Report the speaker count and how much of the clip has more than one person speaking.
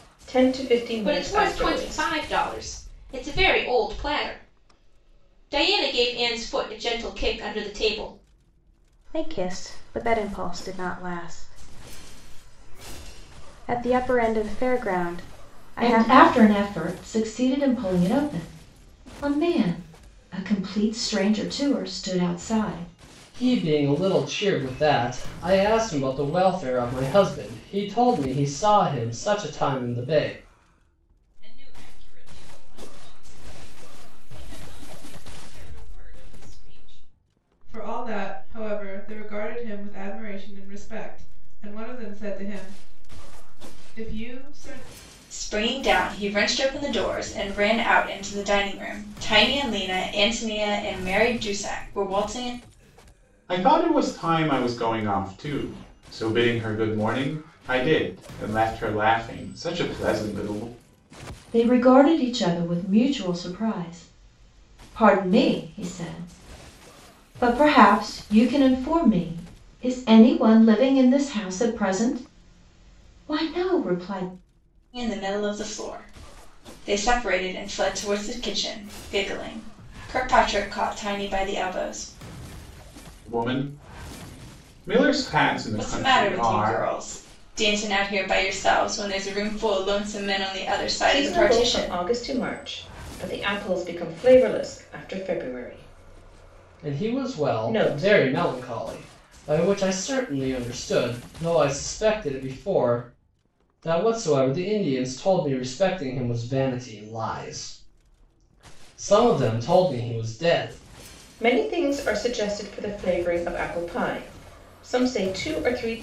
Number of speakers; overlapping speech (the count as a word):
nine, about 4%